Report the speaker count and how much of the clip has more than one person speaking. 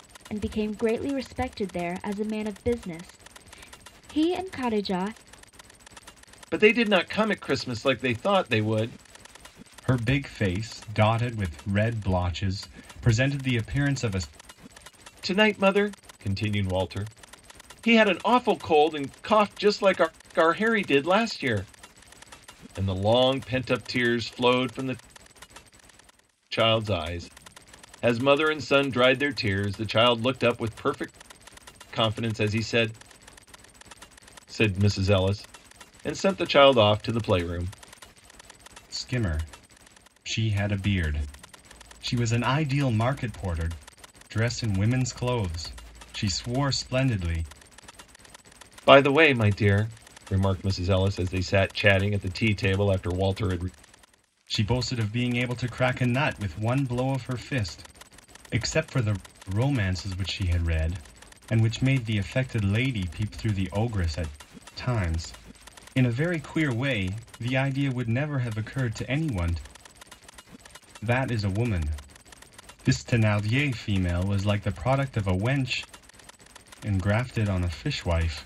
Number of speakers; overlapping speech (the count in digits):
3, no overlap